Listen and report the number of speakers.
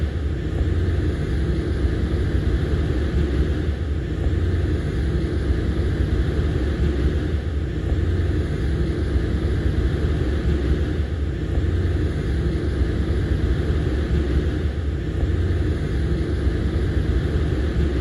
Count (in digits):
0